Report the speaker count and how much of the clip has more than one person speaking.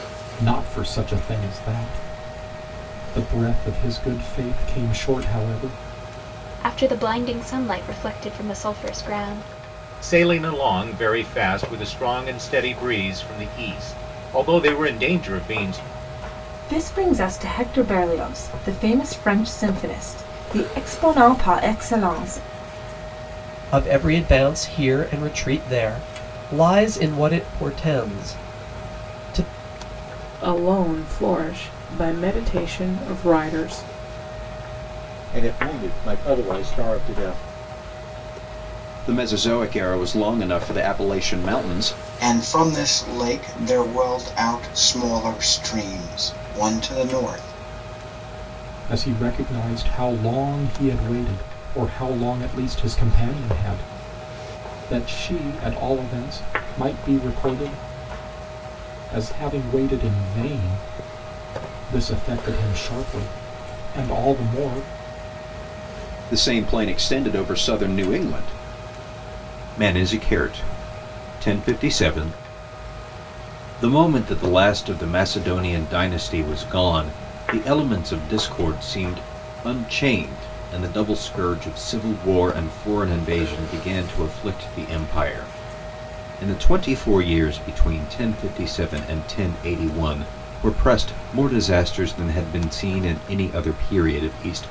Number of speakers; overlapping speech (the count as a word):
nine, no overlap